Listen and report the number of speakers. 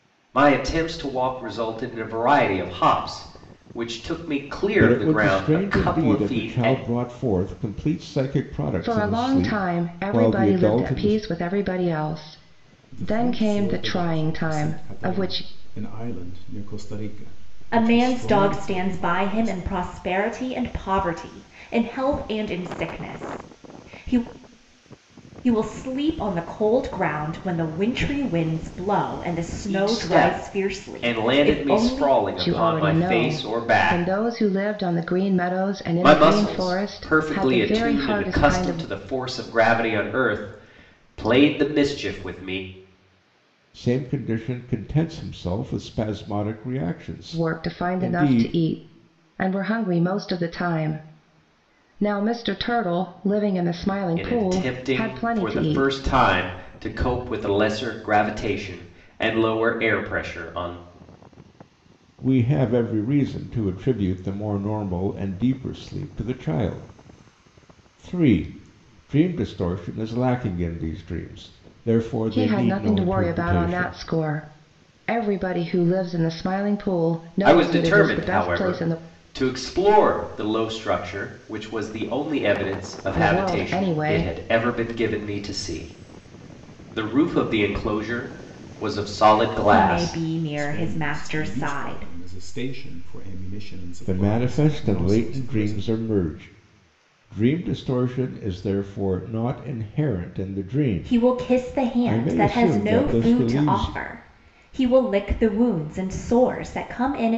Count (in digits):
5